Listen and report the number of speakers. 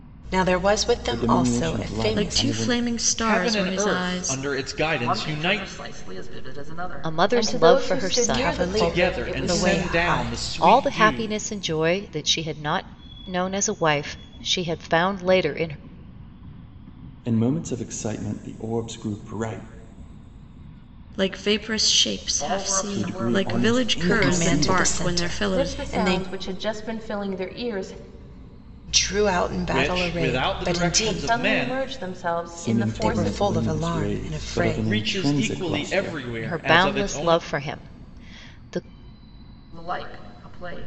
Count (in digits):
7